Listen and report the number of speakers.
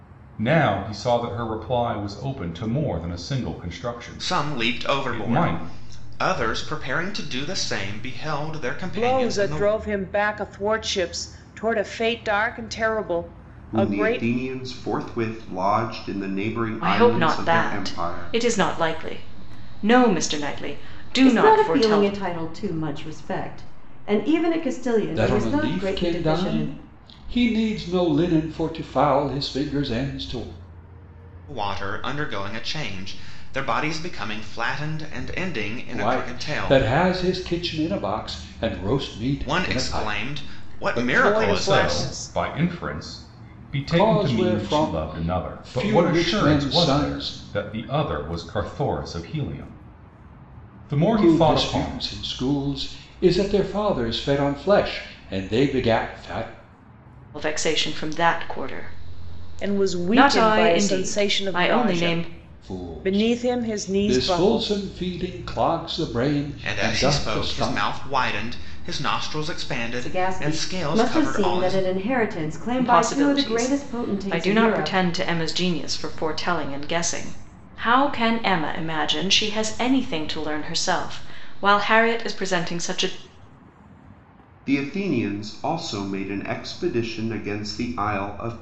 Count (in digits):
7